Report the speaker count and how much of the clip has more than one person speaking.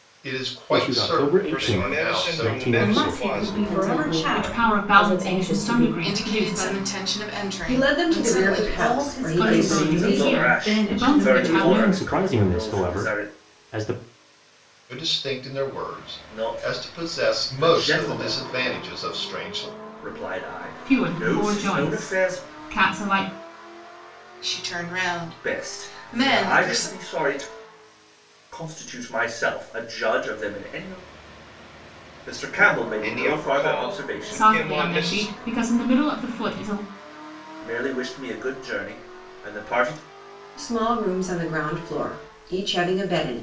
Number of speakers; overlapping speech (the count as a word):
nine, about 45%